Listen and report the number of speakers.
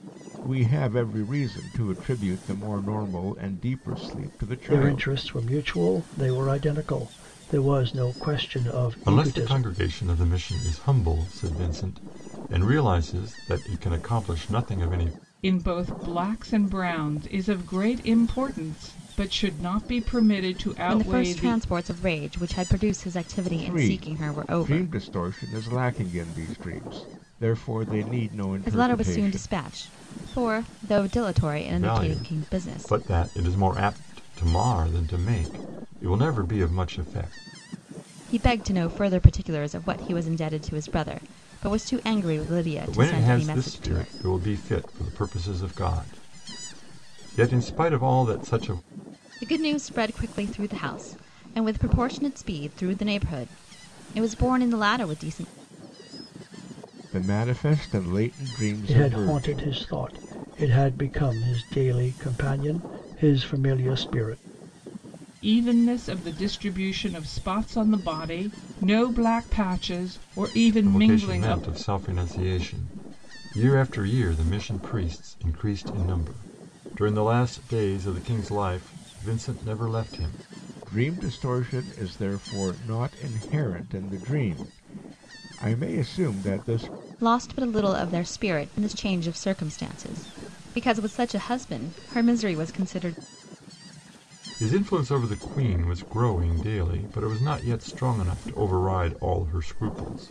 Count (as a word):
five